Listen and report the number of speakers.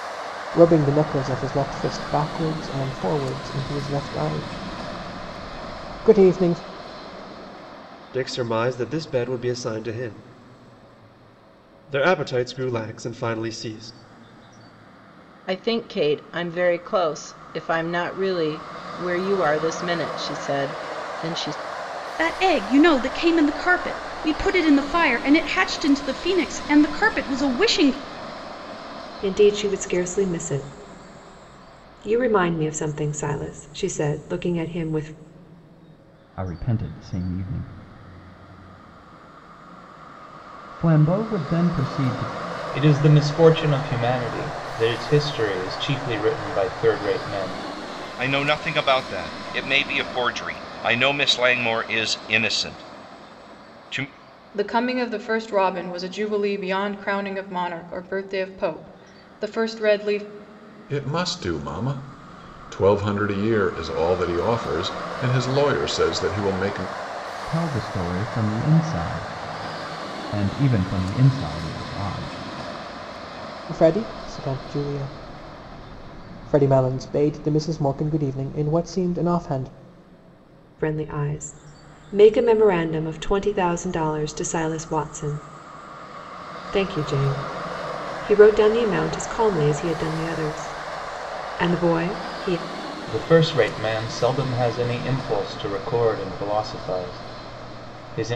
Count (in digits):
10